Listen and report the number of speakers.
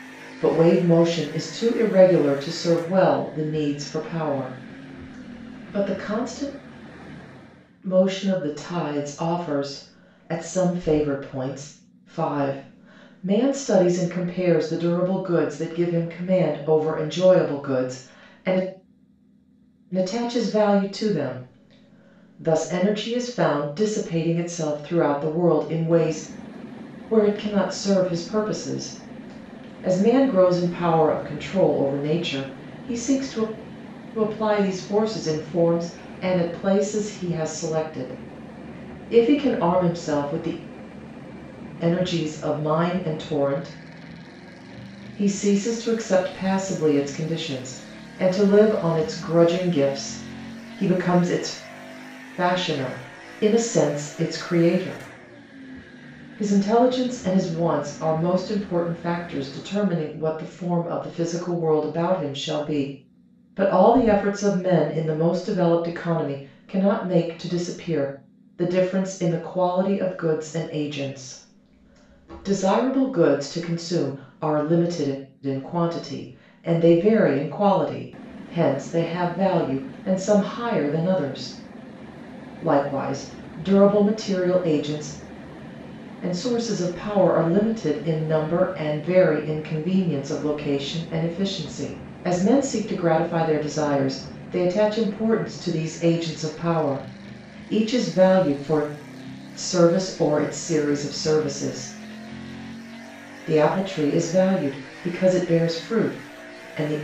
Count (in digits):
1